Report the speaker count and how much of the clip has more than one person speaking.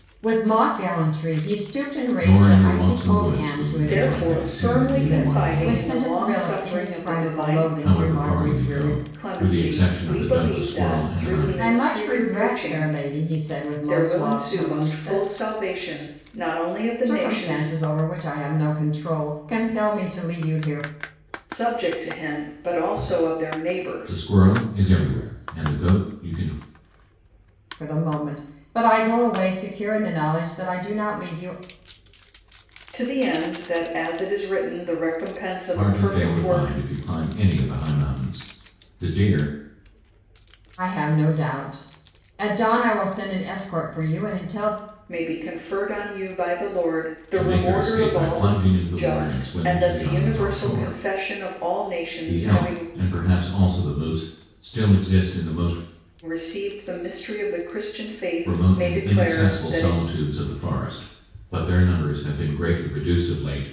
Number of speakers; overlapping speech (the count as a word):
three, about 33%